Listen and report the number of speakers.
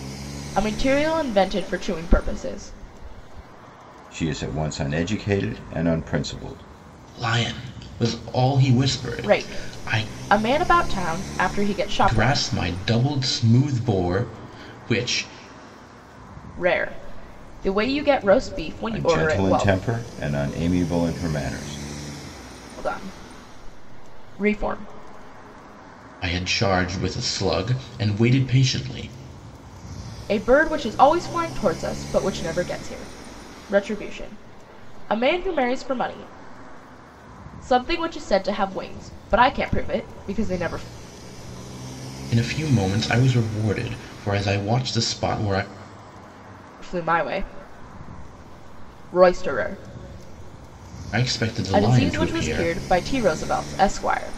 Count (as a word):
three